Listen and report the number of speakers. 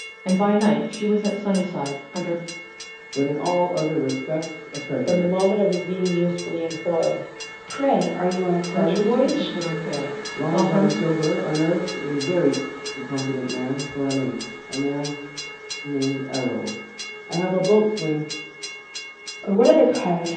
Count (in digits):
4